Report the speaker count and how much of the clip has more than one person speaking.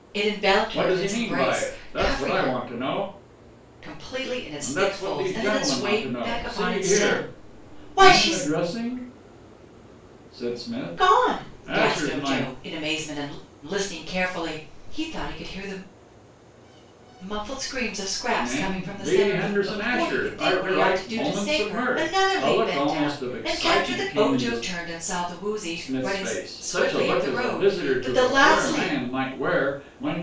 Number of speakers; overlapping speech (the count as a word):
two, about 54%